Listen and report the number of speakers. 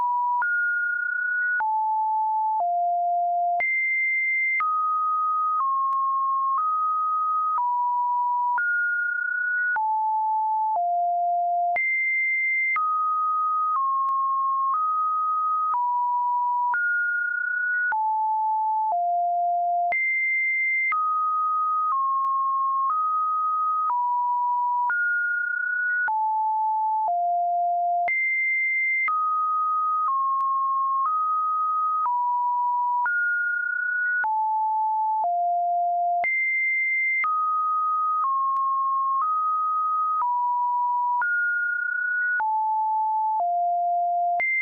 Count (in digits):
0